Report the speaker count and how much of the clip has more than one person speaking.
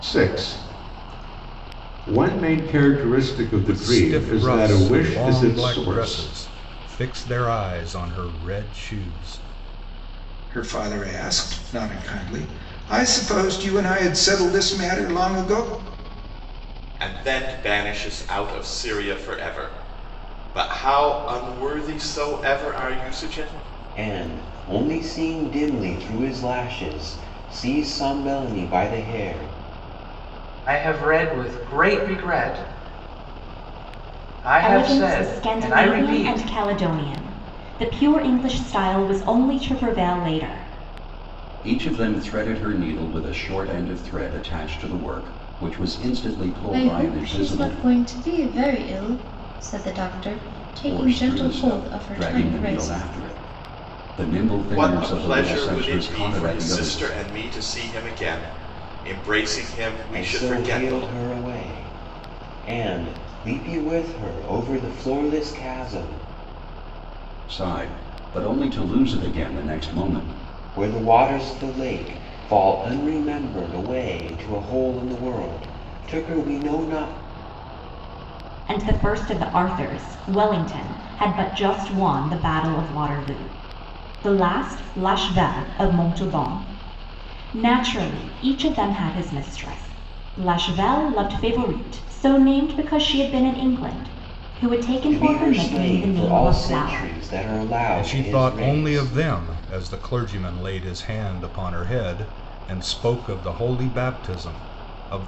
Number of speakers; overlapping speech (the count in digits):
9, about 14%